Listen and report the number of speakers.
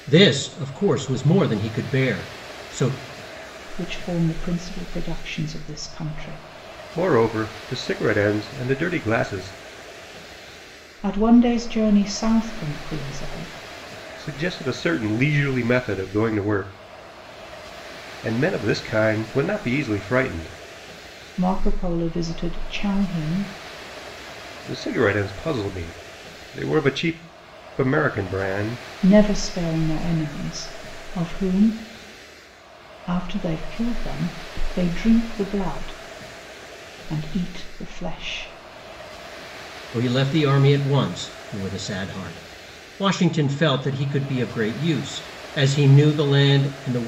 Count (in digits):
3